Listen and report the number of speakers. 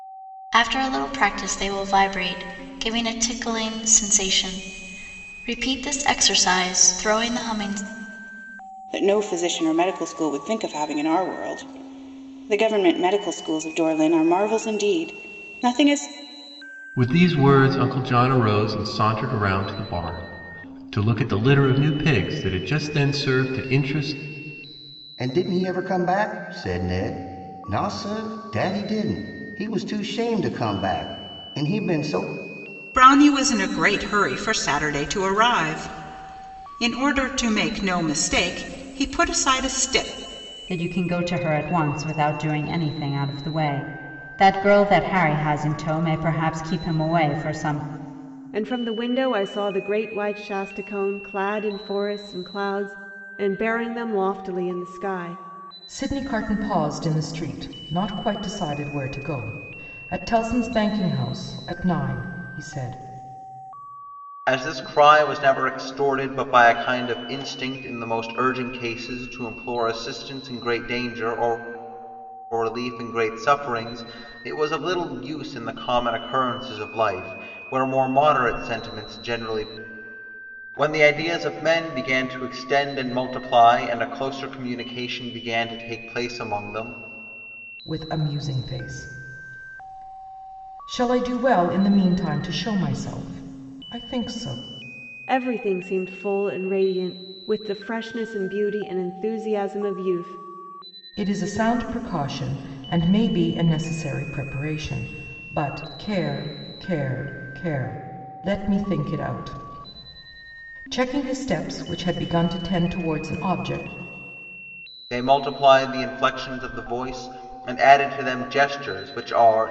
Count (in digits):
9